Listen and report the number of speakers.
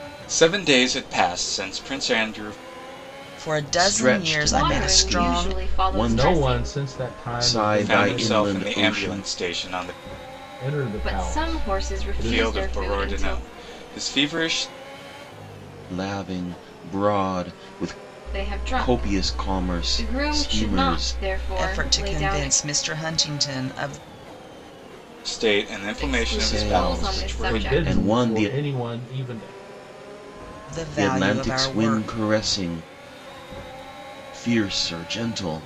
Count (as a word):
five